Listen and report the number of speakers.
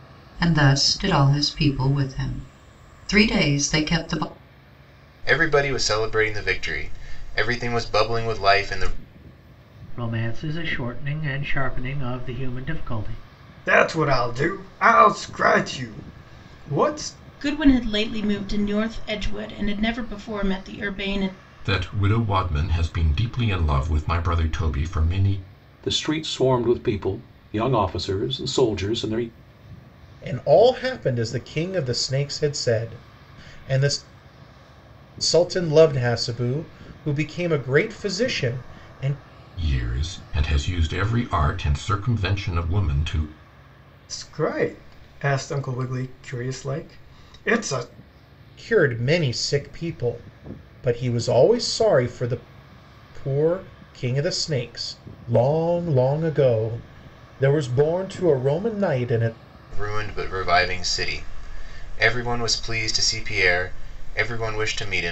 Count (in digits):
8